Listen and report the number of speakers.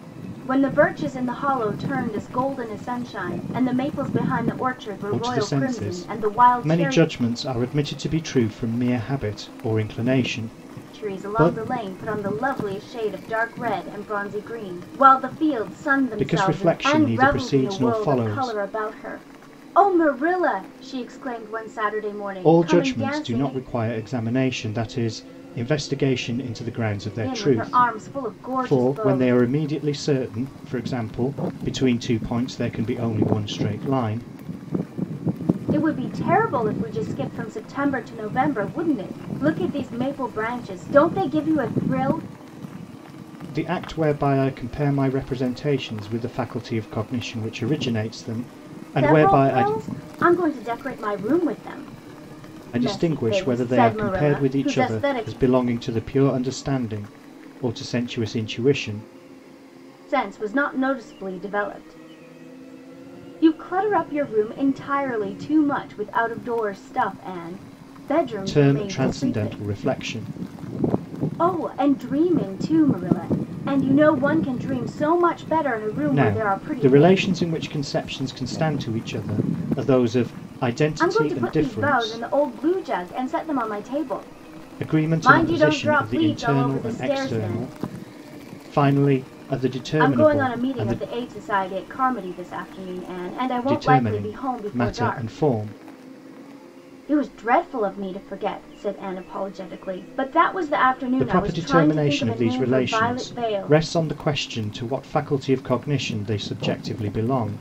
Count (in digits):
2